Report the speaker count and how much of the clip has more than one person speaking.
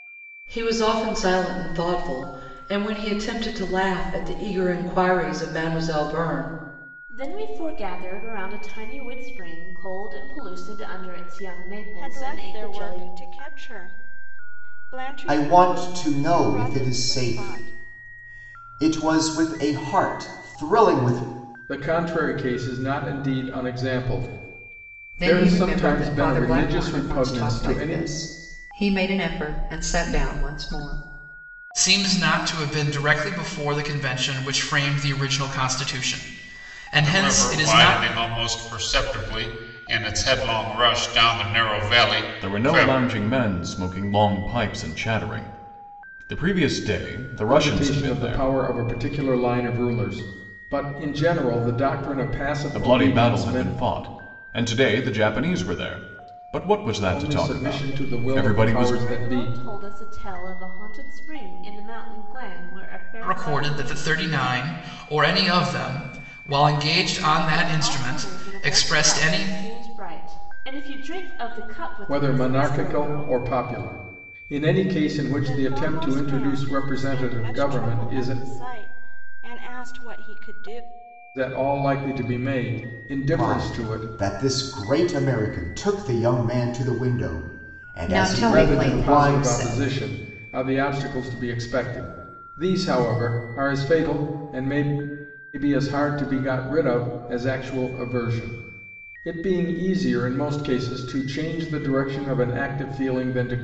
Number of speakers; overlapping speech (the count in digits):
9, about 22%